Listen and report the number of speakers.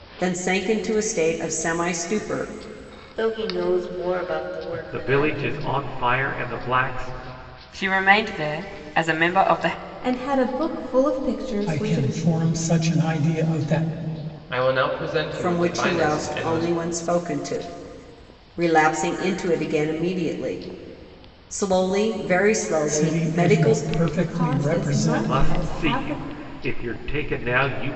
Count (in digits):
7